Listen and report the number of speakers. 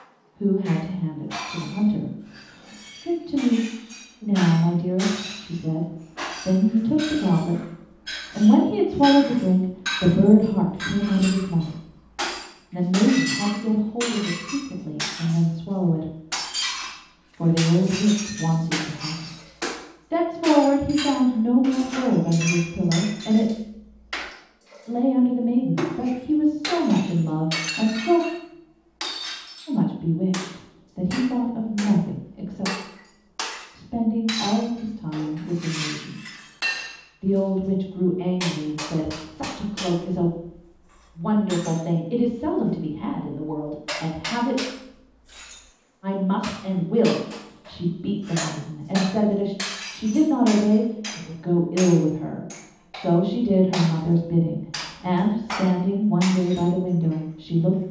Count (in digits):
1